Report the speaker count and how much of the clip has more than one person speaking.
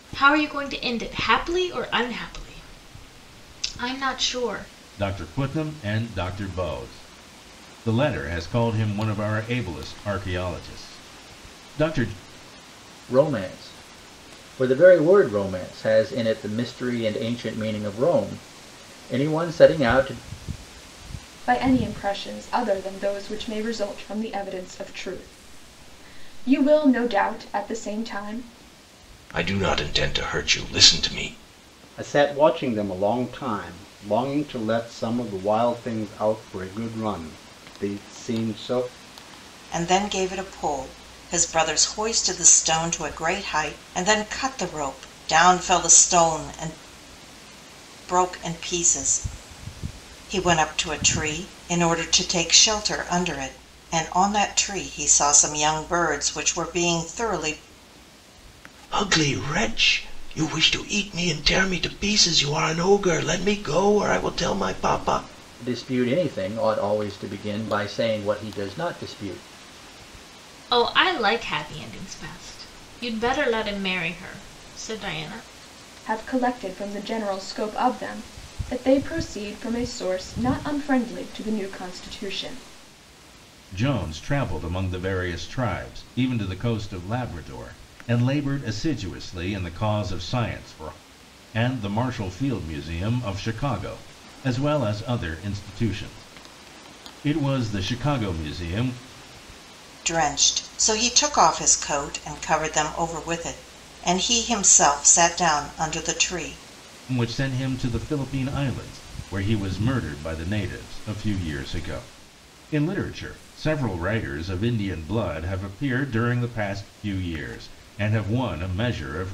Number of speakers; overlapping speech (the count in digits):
7, no overlap